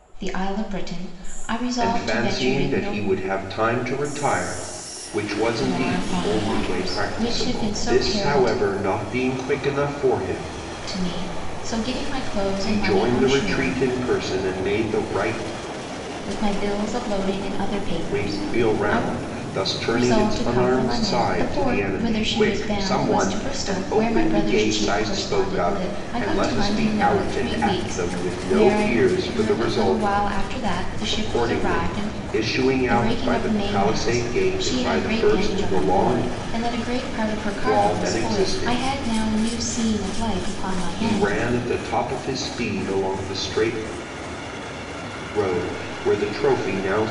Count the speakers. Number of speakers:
2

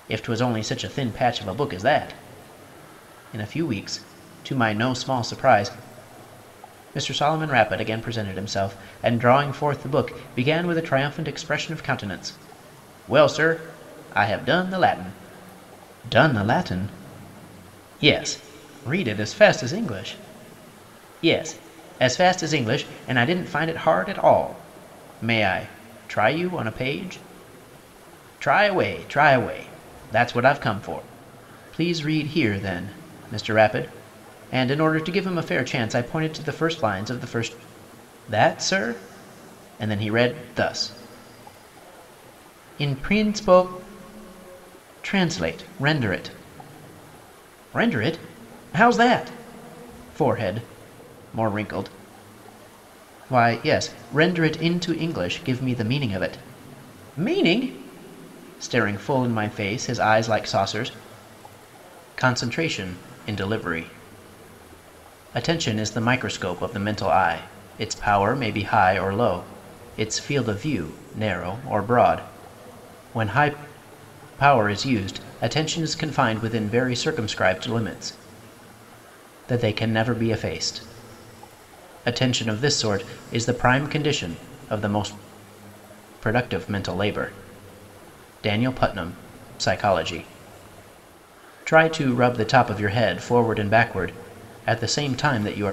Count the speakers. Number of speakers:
1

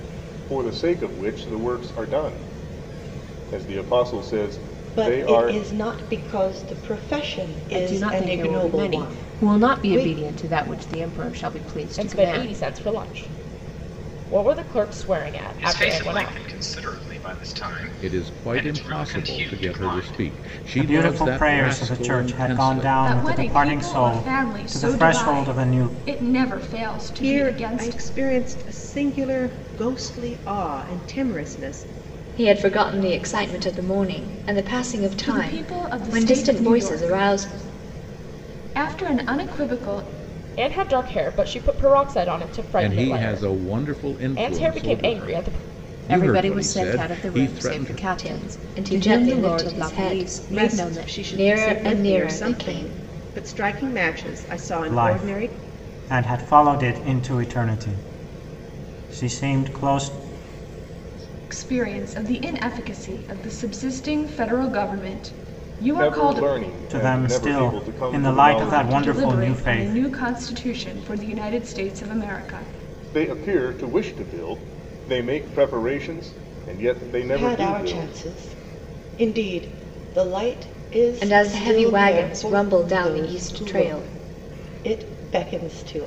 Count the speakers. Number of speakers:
10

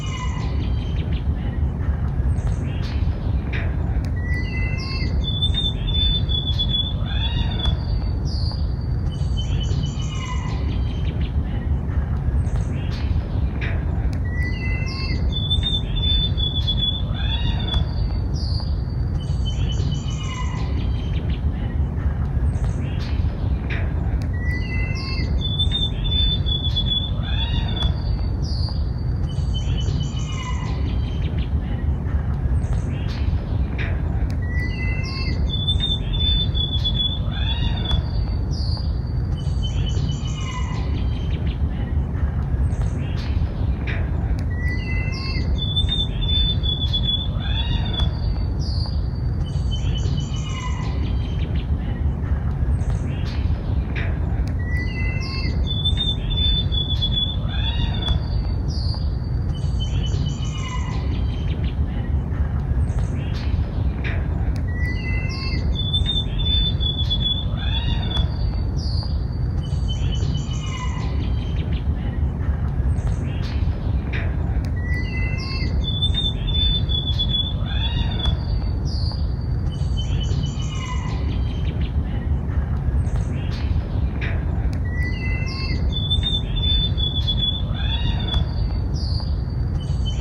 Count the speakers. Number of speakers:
0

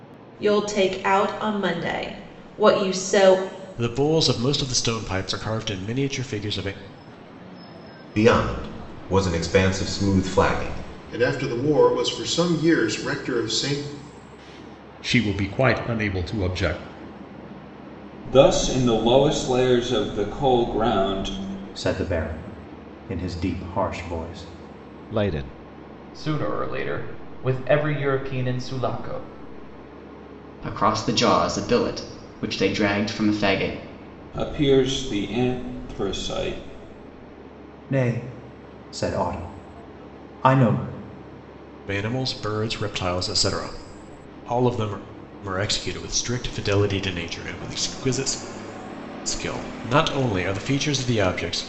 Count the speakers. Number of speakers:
10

